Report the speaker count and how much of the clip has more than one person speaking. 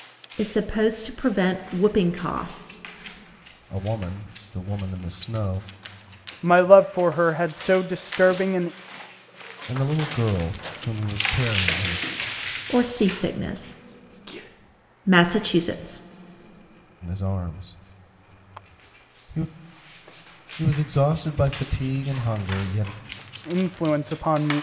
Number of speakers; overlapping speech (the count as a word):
three, no overlap